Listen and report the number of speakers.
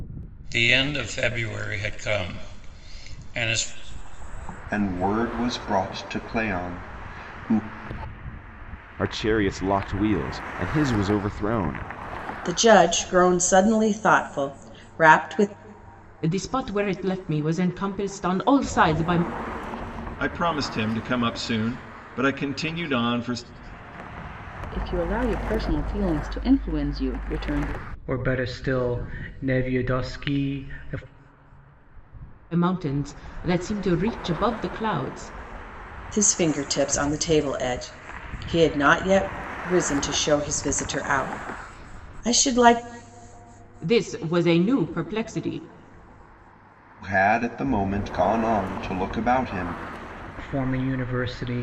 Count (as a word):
eight